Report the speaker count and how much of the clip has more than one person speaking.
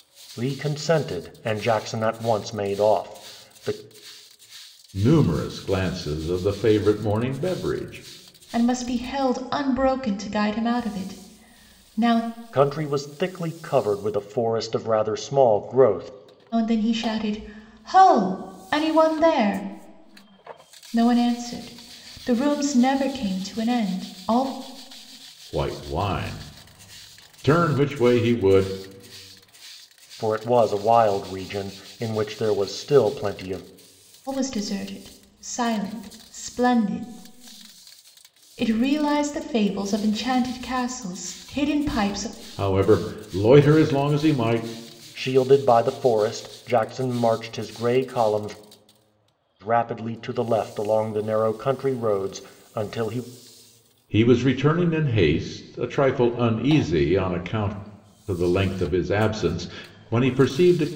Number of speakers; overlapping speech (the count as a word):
three, no overlap